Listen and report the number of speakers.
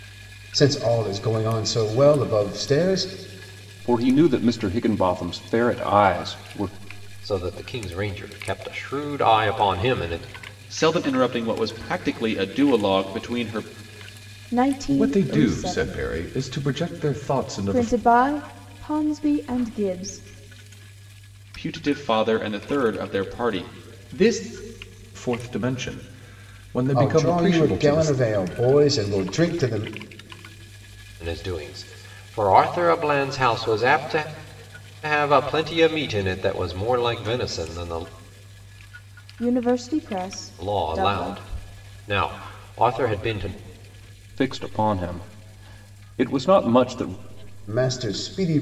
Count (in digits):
6